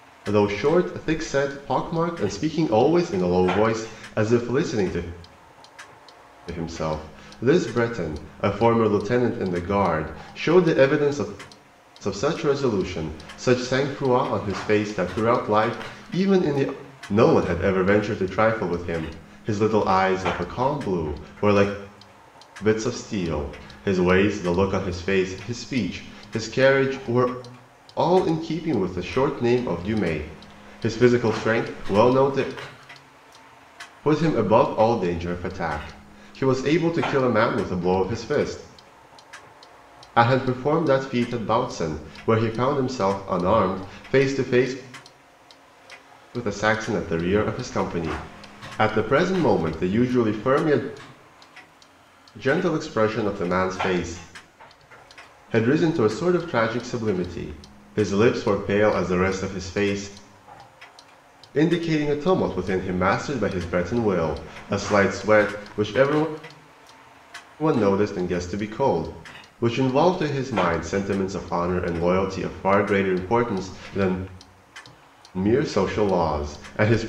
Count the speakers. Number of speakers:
one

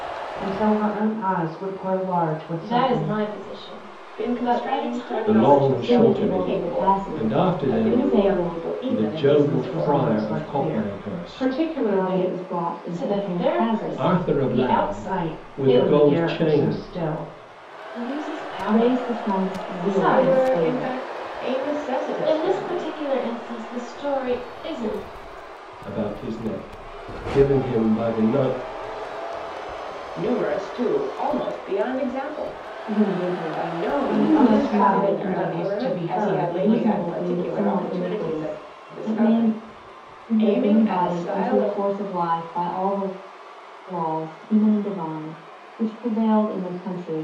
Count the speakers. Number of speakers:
five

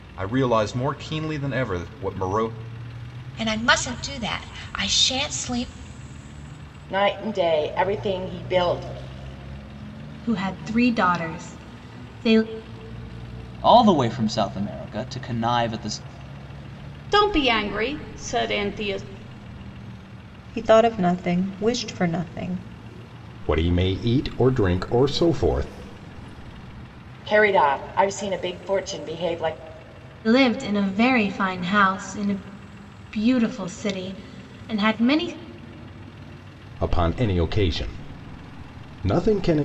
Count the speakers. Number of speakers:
eight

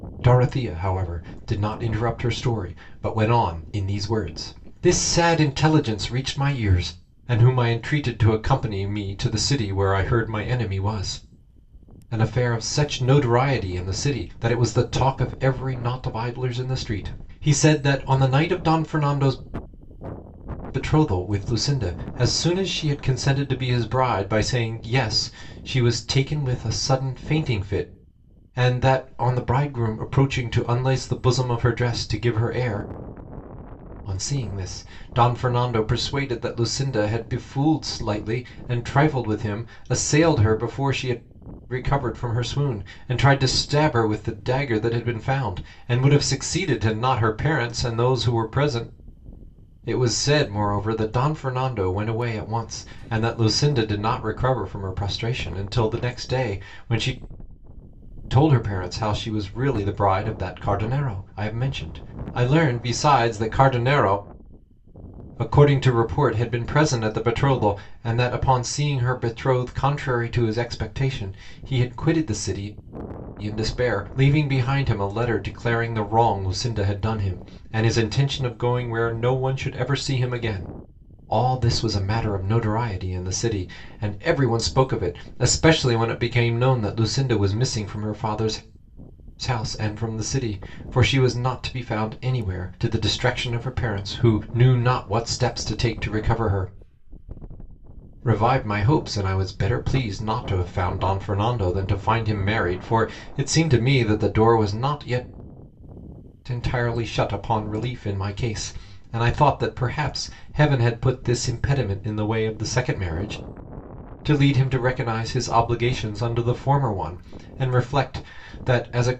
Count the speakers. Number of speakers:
one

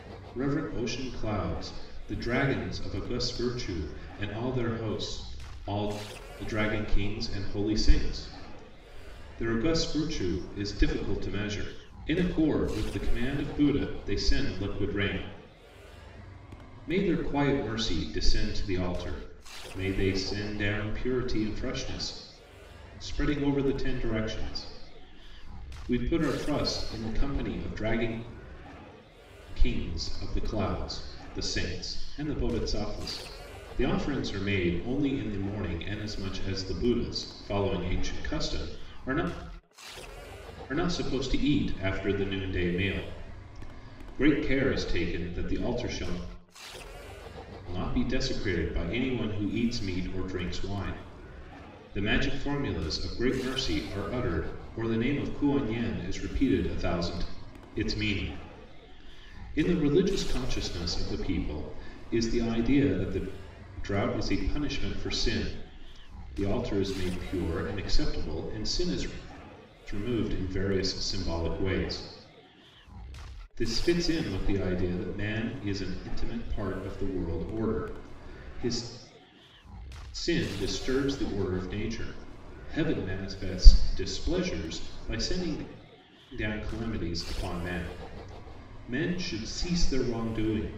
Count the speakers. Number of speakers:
one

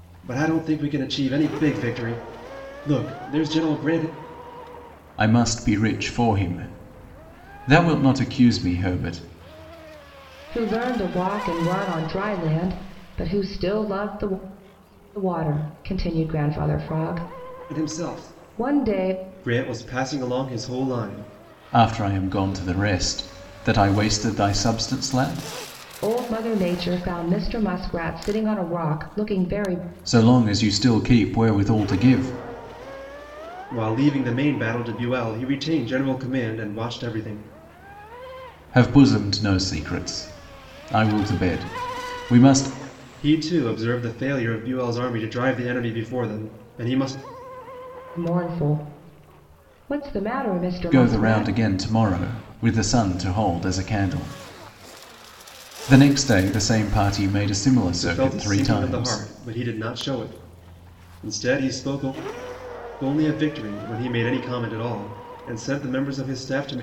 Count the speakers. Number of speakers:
three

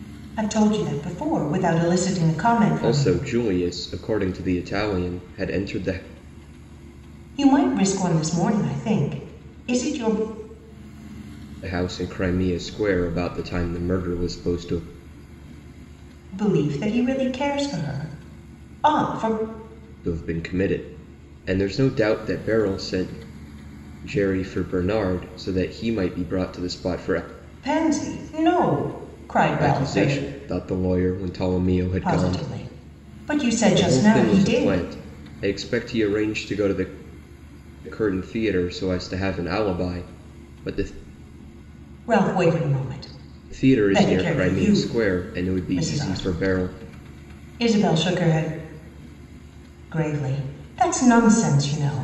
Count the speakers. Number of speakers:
two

